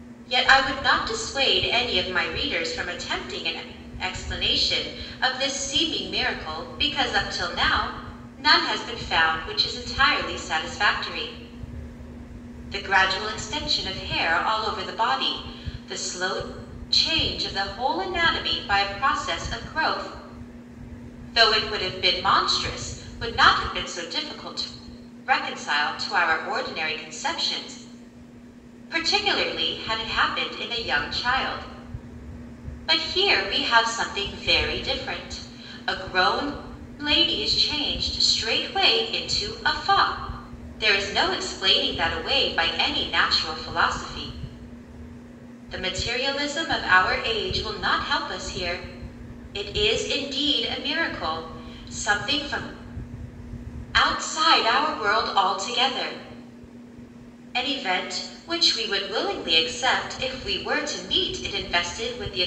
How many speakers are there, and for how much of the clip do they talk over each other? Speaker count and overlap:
one, no overlap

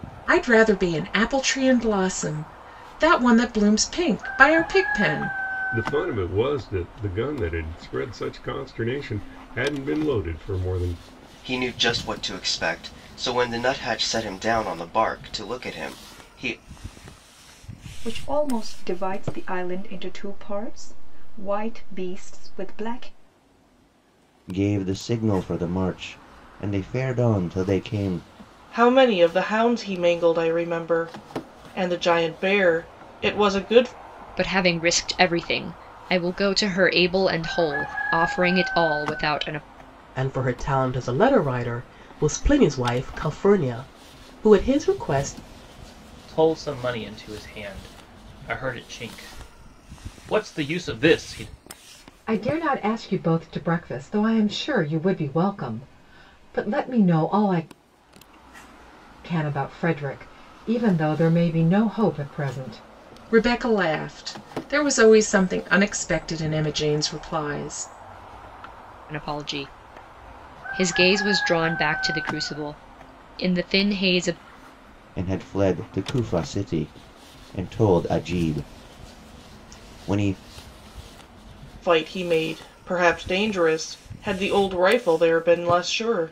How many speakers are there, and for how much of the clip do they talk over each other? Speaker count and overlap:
ten, no overlap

